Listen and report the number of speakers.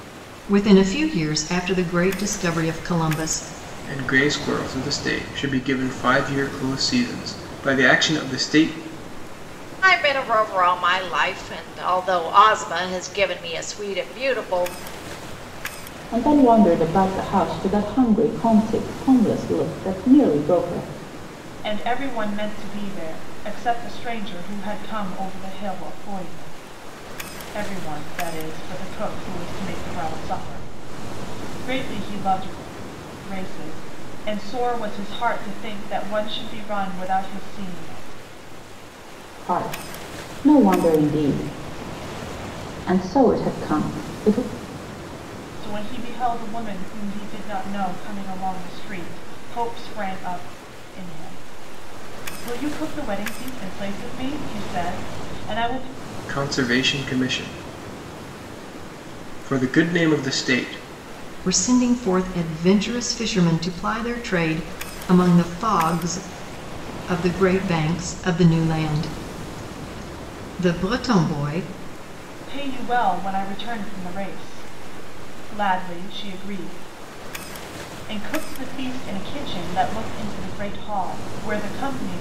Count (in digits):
5